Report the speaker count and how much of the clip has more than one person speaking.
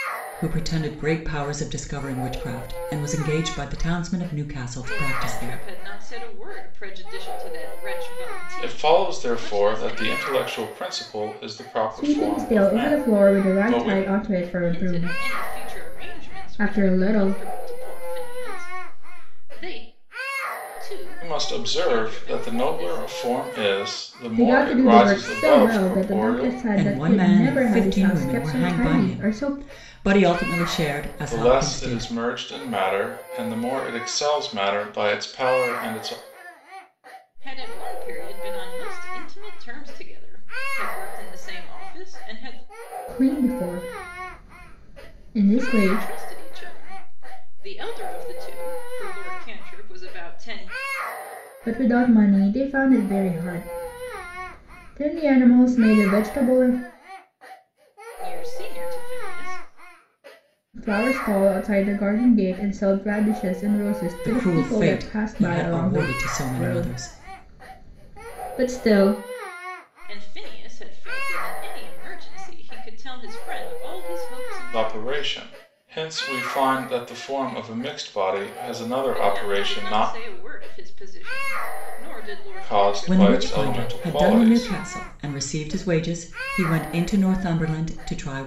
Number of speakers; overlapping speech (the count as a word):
four, about 25%